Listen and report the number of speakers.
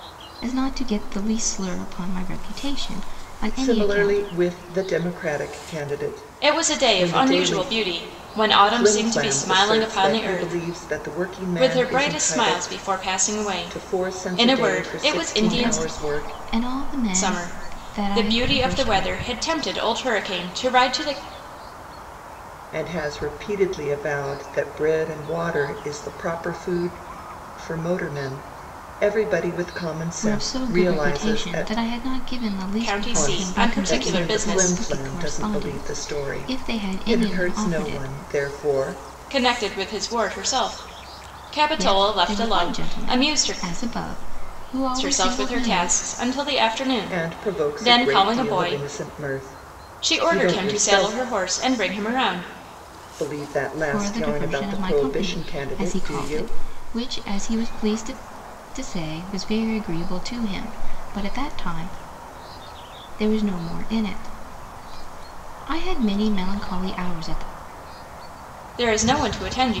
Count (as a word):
three